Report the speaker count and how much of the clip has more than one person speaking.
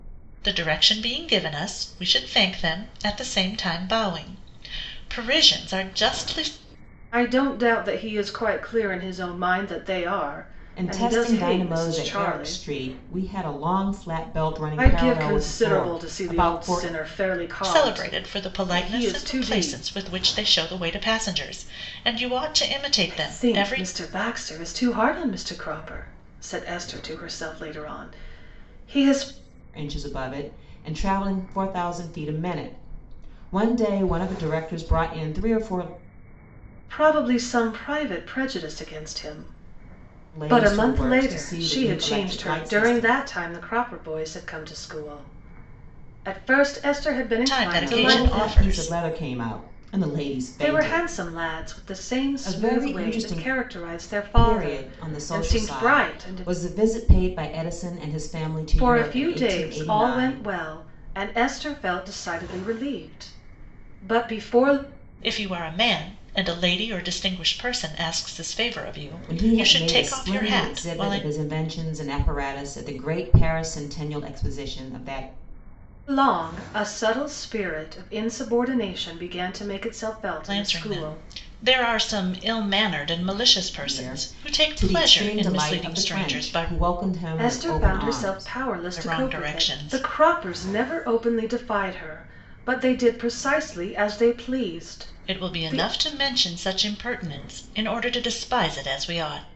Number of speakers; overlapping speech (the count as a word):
three, about 27%